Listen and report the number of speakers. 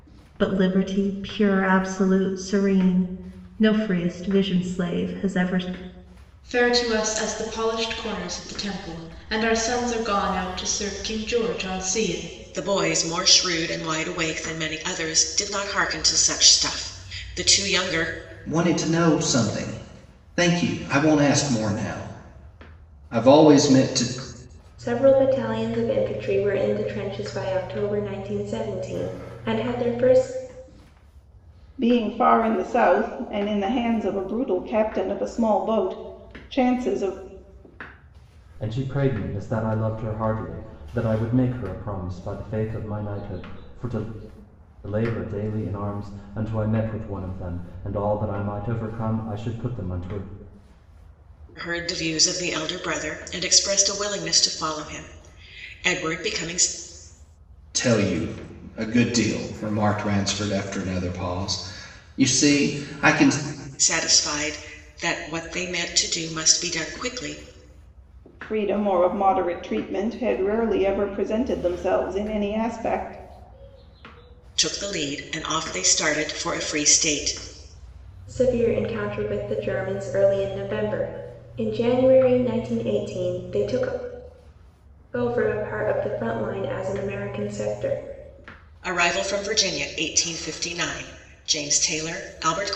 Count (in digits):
7